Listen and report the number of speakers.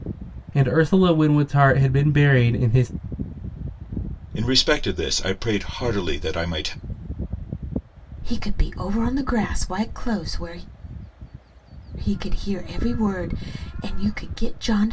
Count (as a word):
three